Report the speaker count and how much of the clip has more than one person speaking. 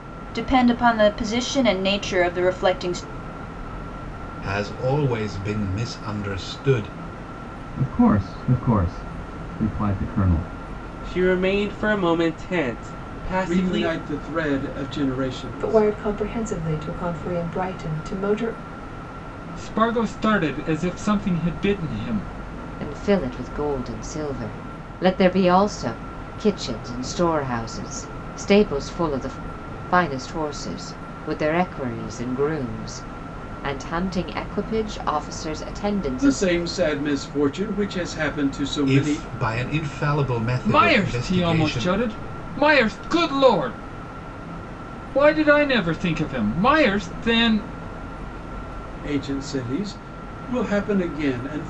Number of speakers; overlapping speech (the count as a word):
eight, about 5%